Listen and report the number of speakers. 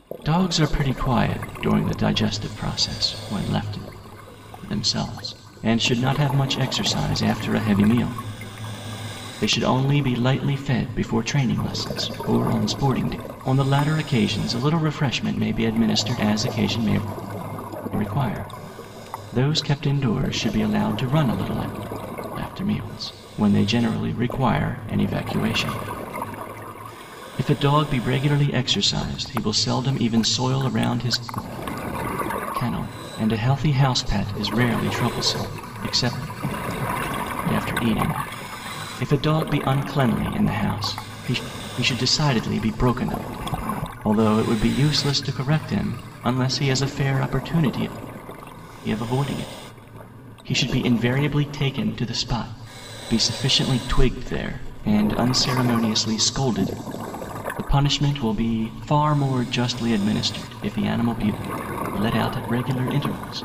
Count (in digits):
1